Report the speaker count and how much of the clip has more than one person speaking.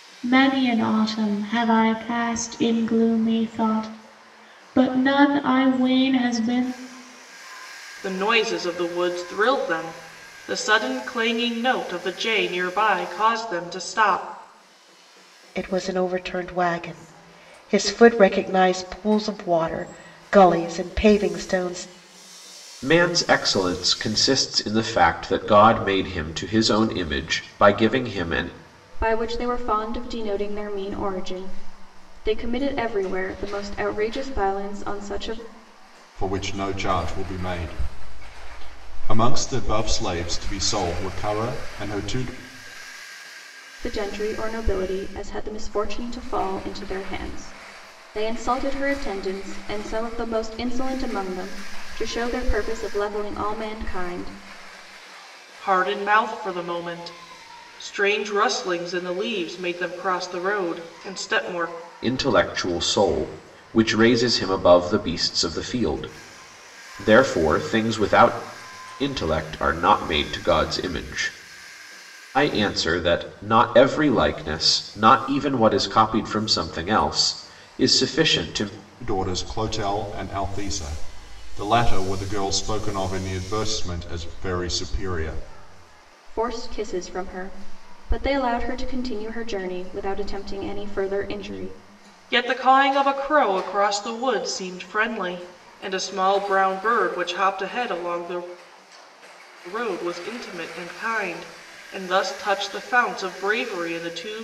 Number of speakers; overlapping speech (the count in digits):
6, no overlap